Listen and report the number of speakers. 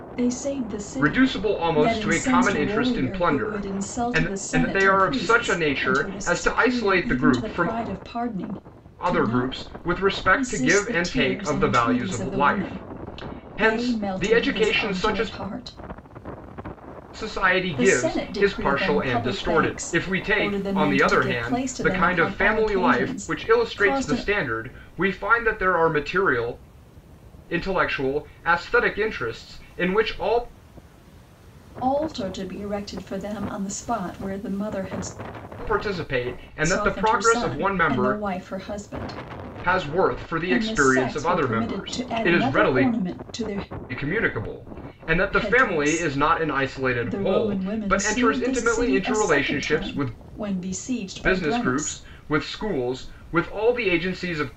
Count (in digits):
2